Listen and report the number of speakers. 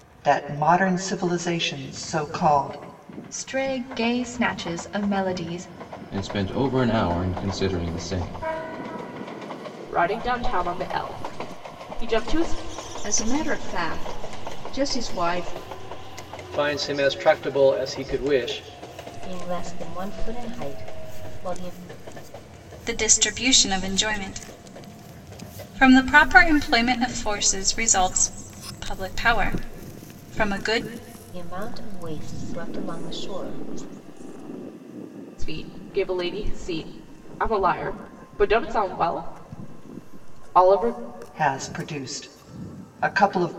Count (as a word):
eight